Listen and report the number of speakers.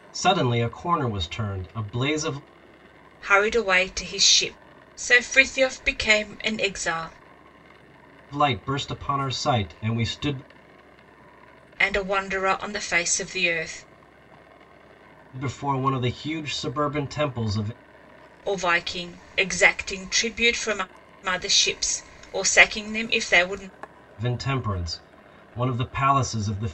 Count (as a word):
two